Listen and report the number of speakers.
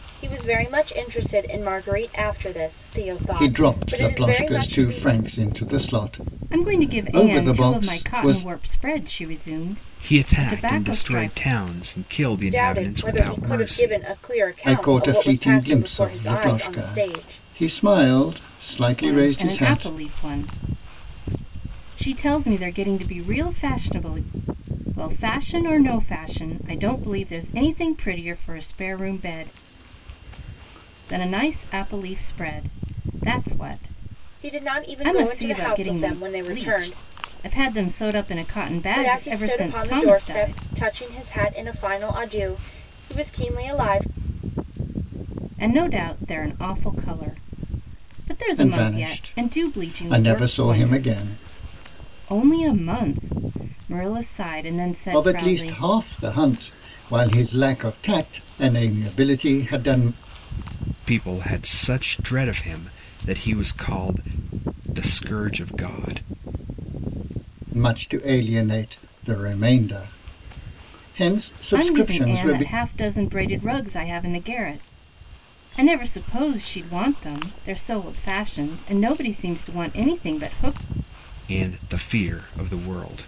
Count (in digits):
4